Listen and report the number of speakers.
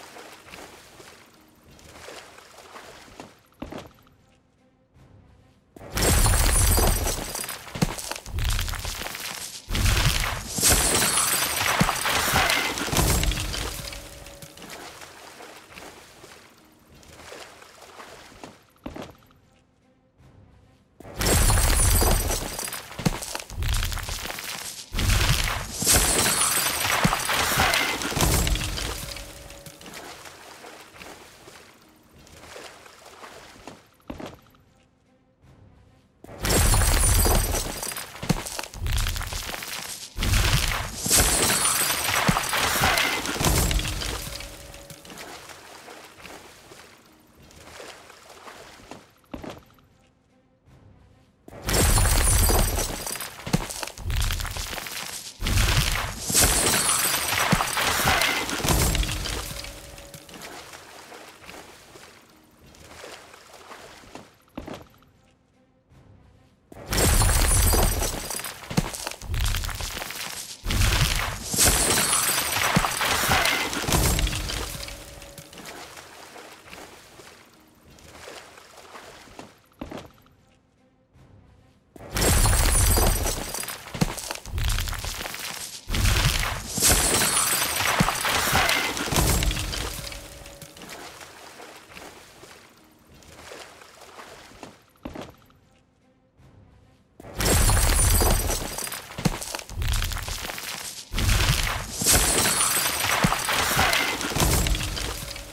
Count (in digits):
0